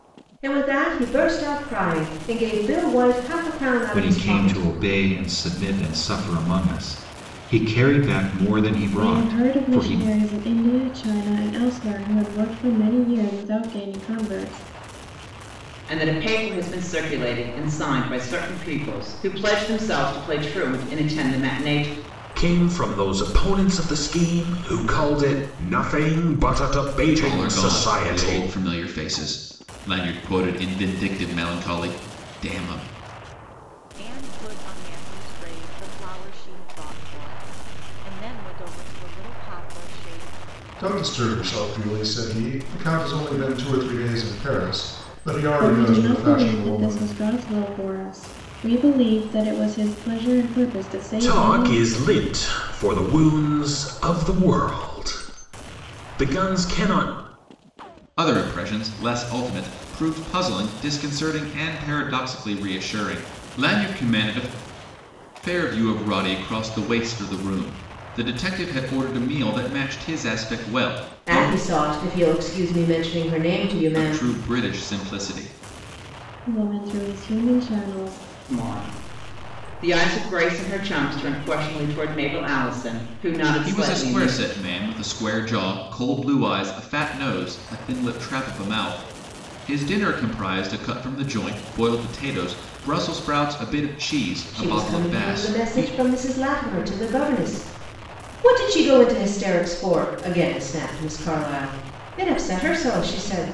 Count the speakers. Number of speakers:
8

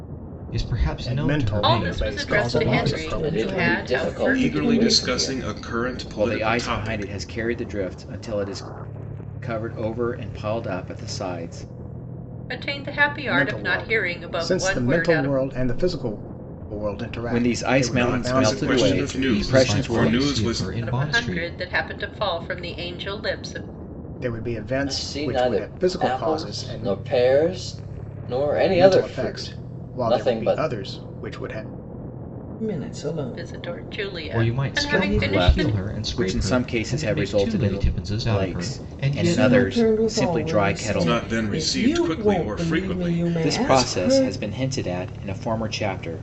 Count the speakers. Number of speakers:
7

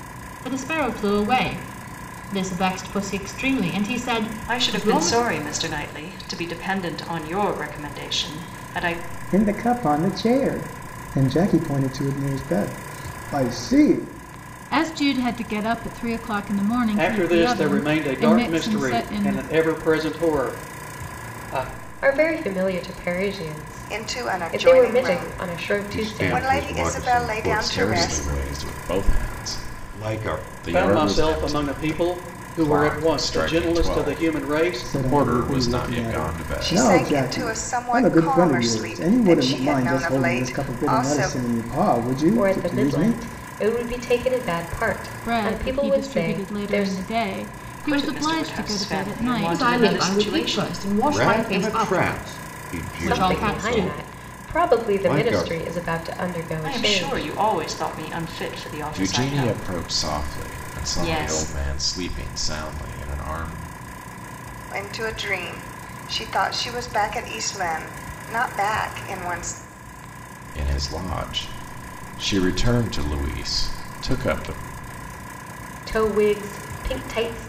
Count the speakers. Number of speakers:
9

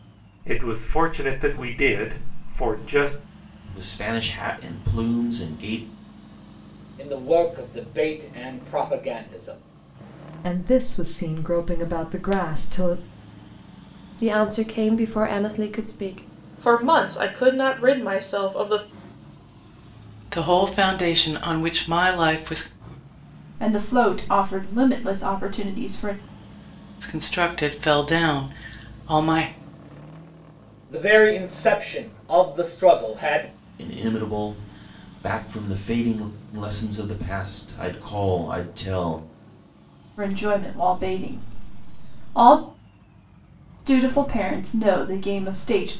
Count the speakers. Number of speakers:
8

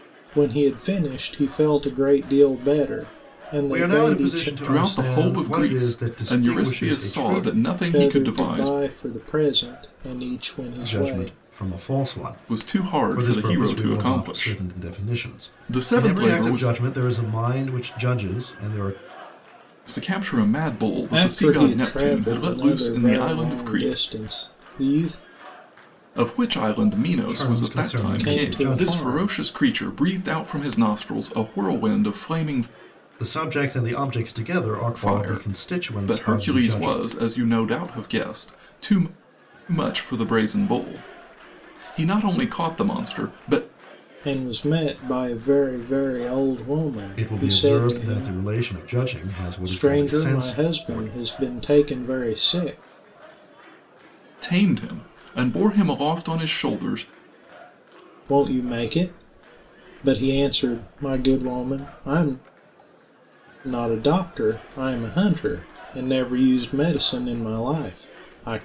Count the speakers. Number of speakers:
3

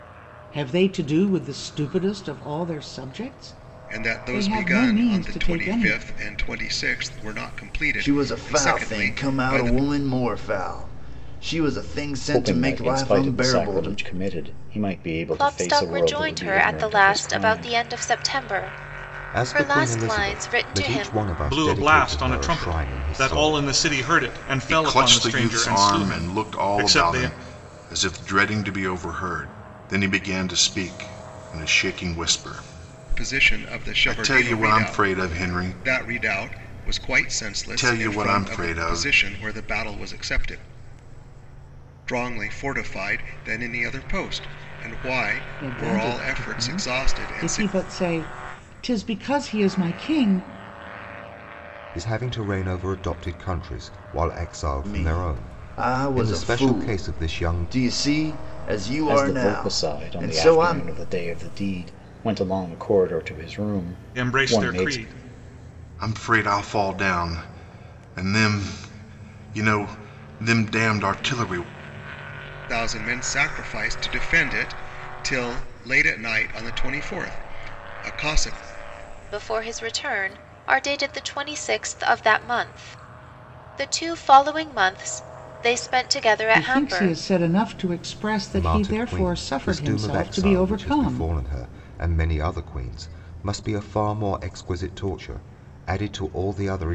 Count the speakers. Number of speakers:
8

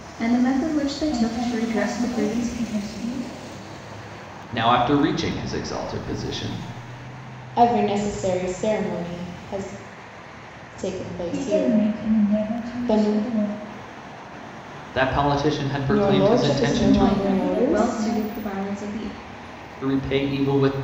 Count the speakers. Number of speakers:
4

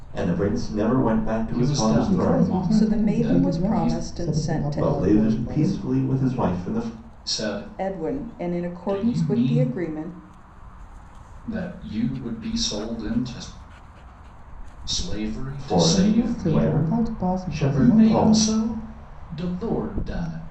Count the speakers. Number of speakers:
4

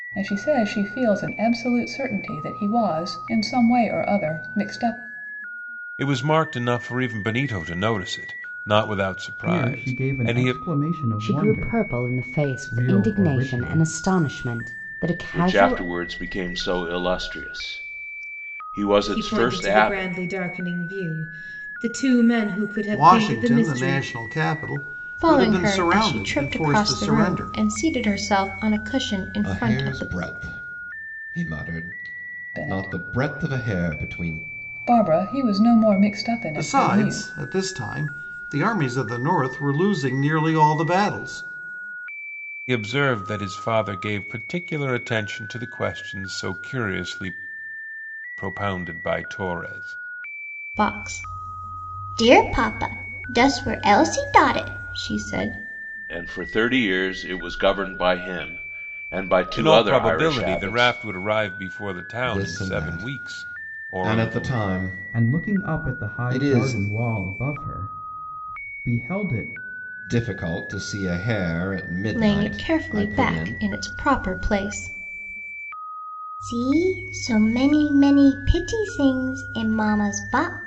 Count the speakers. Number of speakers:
9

